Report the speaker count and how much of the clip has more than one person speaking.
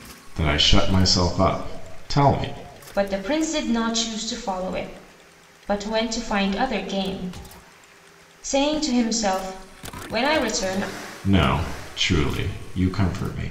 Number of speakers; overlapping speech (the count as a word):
two, no overlap